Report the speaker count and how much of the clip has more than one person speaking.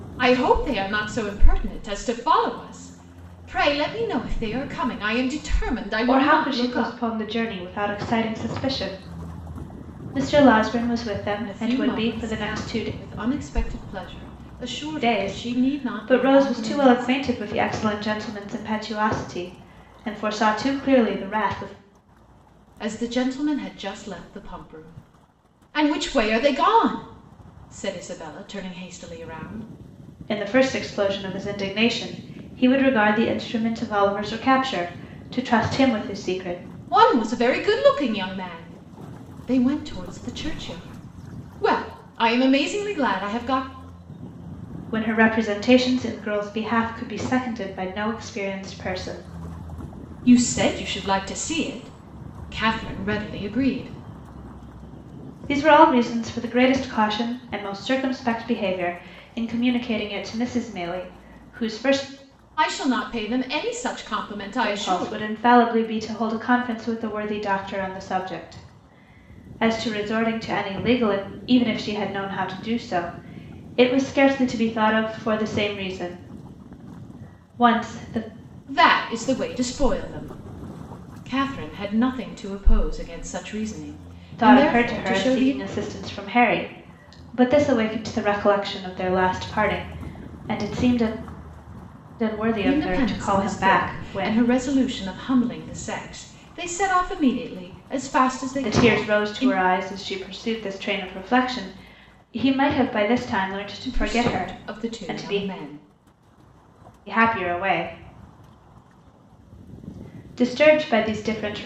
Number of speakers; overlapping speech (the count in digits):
2, about 10%